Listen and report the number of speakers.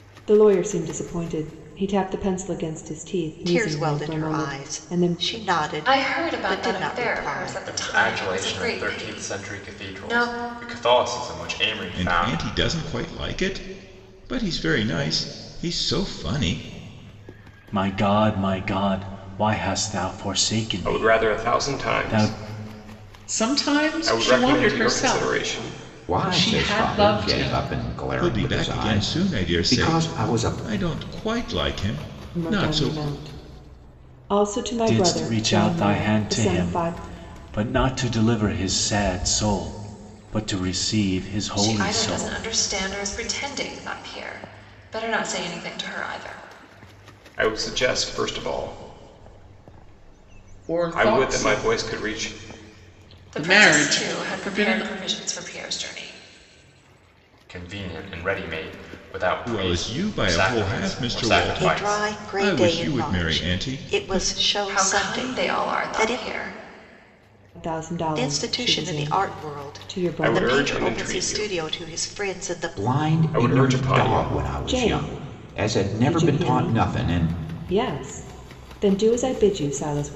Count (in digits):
9